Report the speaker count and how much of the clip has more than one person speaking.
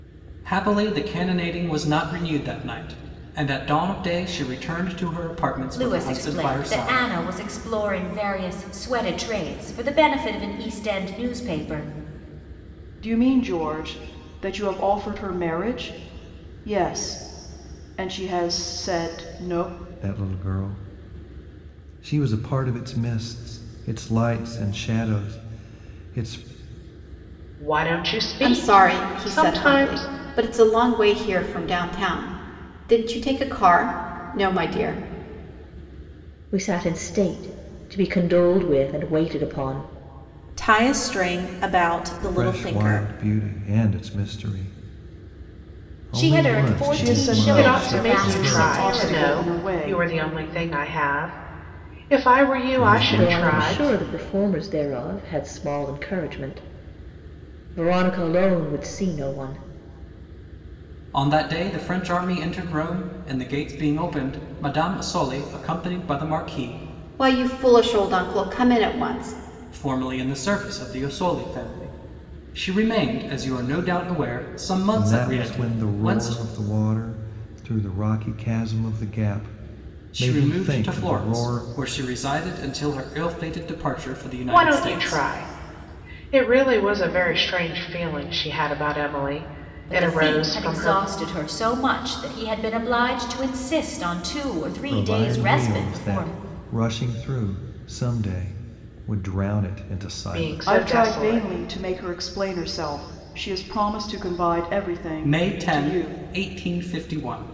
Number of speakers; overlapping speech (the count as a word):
eight, about 17%